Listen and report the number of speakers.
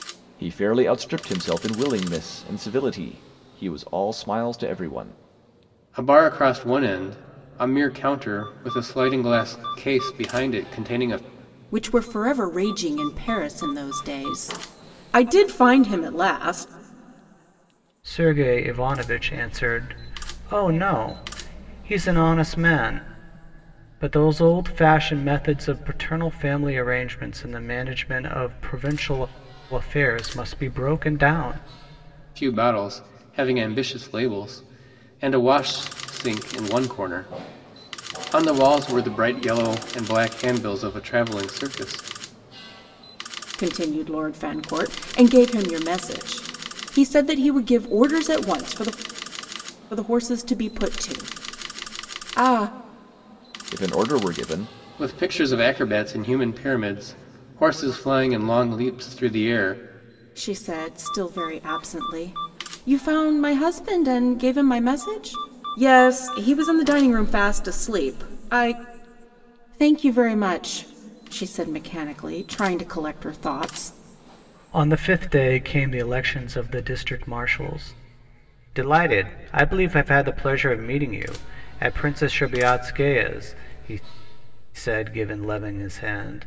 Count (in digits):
4